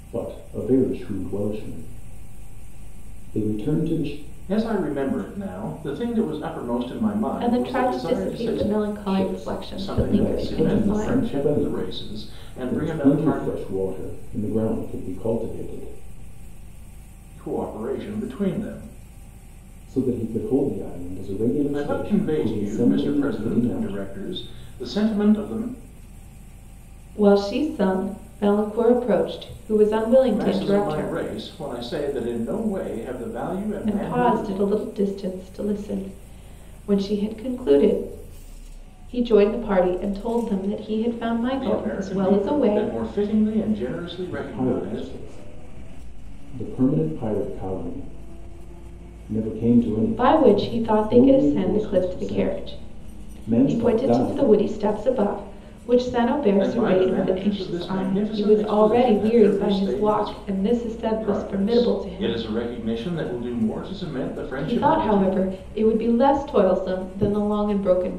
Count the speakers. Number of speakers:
3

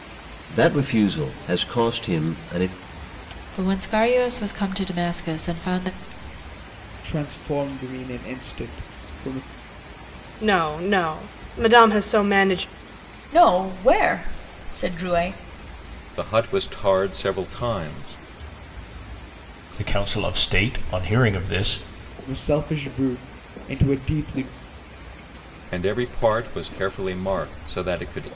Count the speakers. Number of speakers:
7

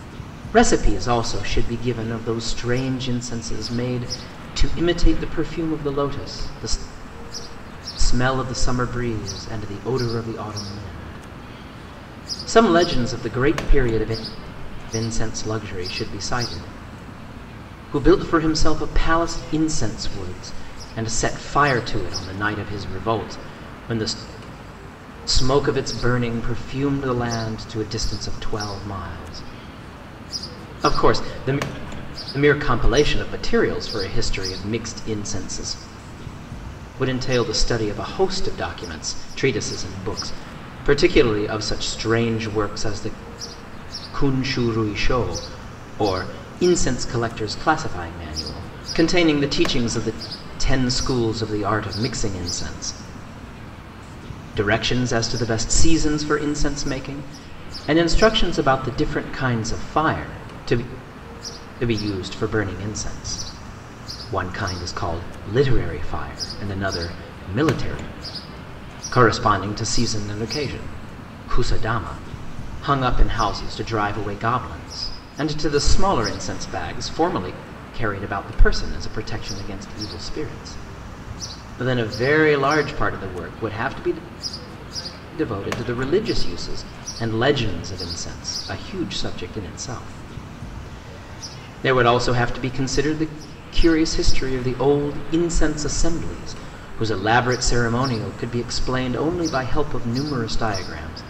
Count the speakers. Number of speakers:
1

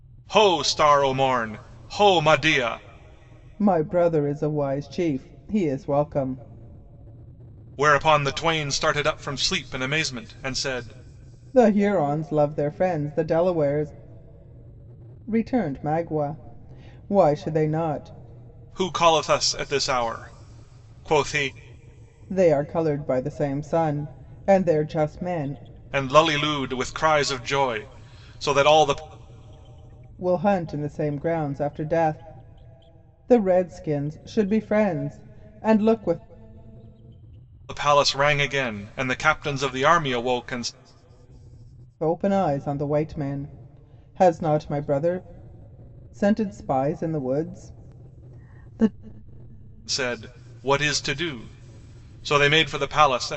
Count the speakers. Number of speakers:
2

